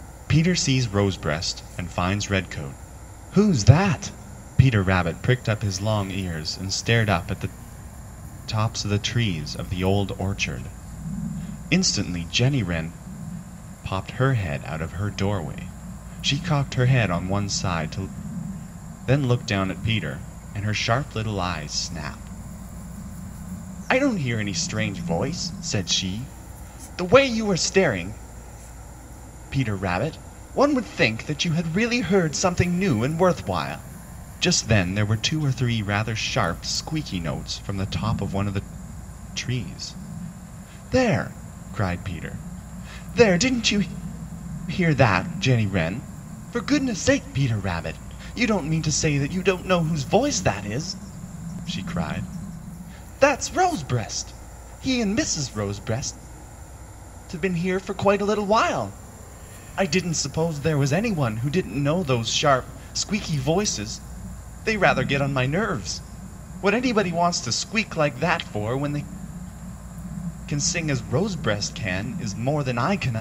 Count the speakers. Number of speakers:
1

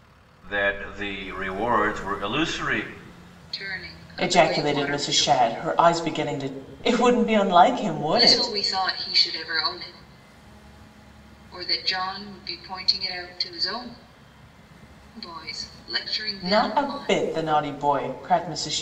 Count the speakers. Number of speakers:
3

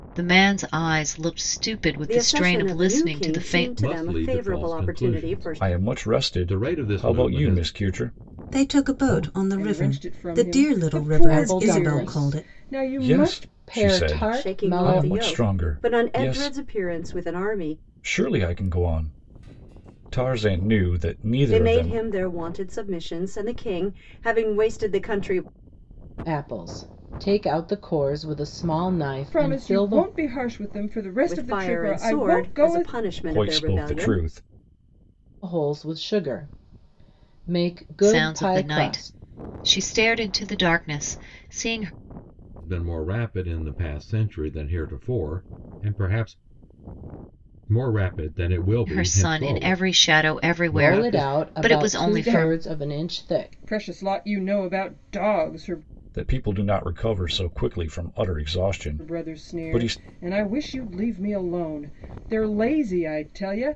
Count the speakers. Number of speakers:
7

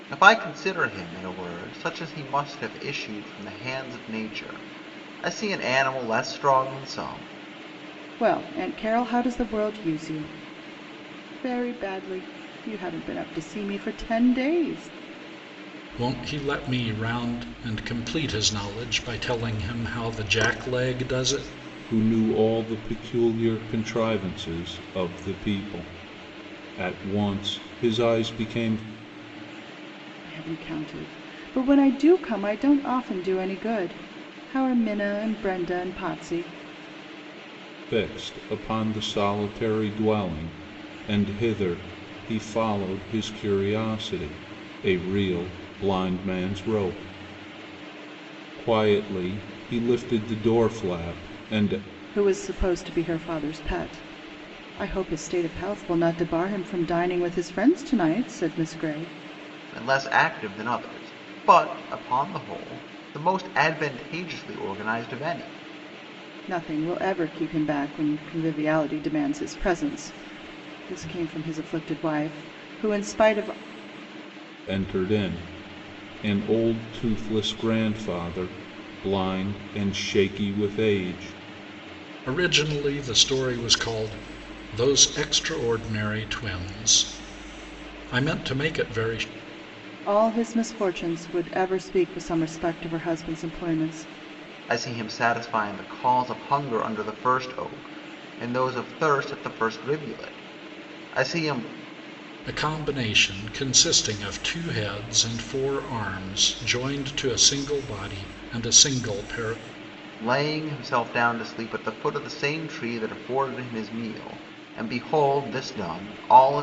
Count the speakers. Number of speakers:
4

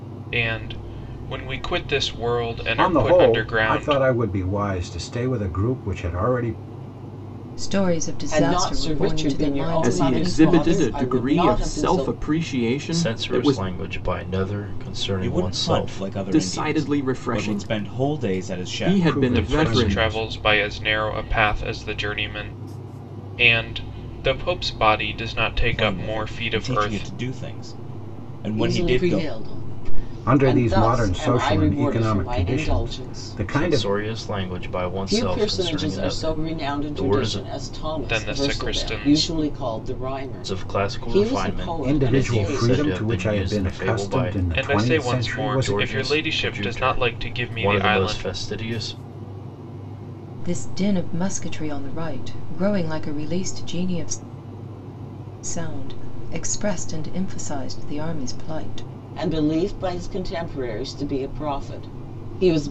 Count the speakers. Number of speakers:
7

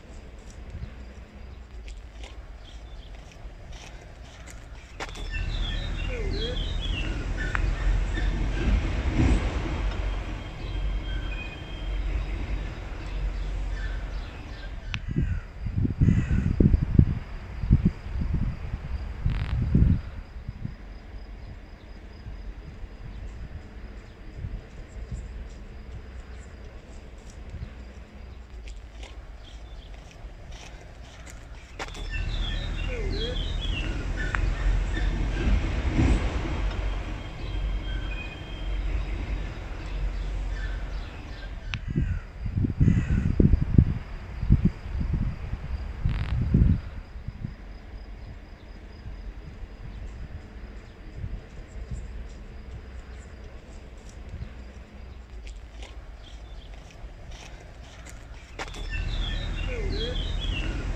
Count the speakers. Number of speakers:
0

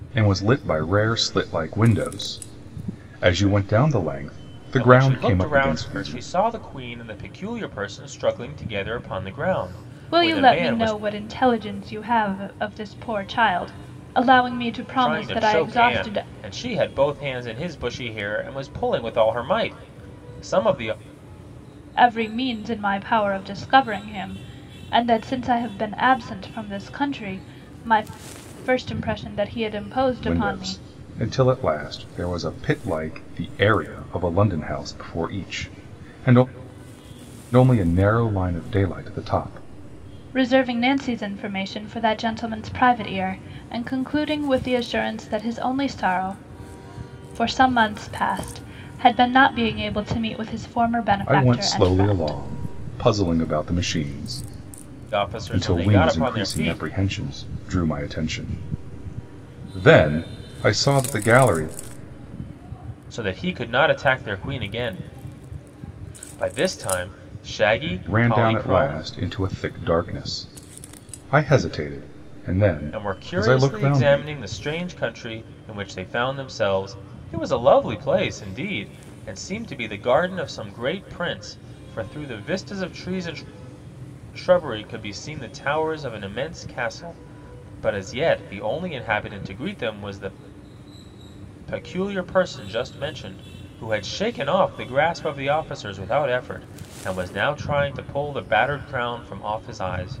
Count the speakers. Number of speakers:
3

